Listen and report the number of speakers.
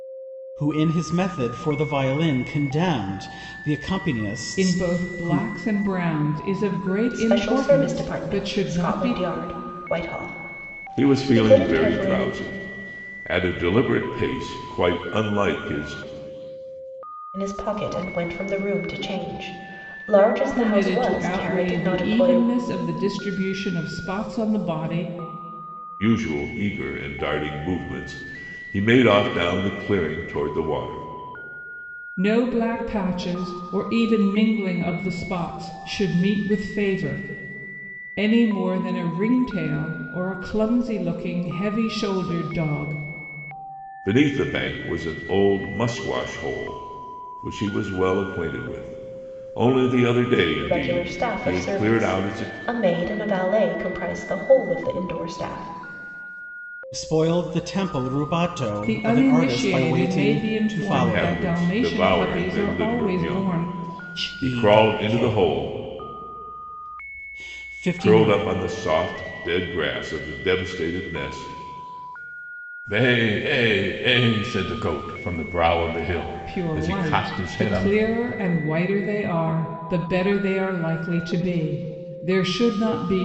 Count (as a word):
four